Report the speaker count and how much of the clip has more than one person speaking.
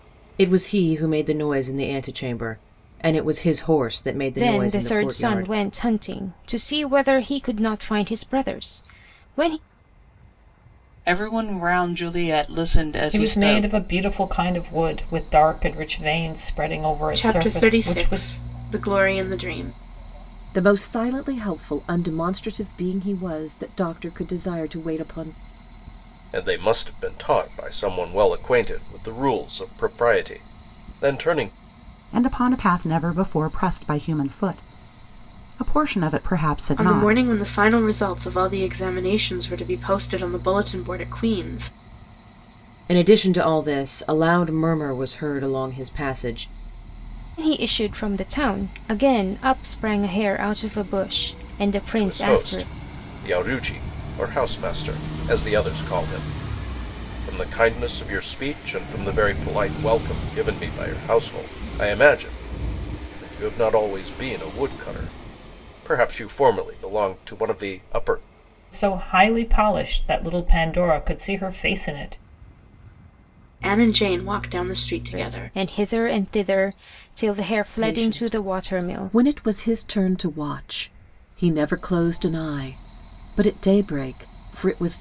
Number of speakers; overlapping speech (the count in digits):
8, about 7%